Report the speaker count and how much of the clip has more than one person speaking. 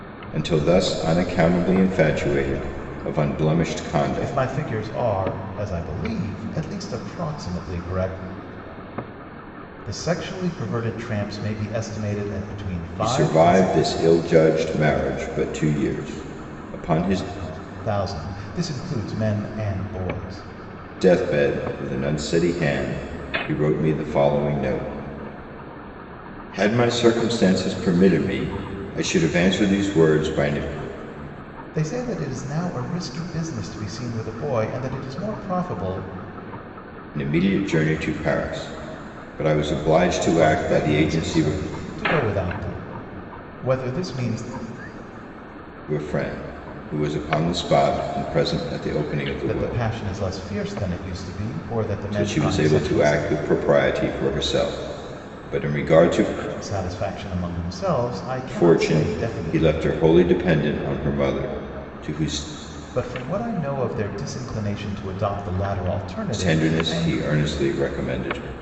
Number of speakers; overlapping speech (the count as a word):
two, about 9%